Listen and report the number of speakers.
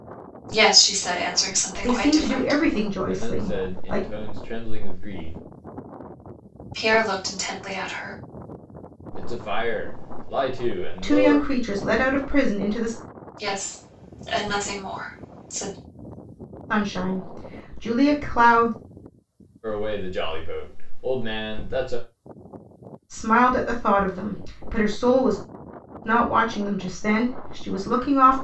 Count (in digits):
3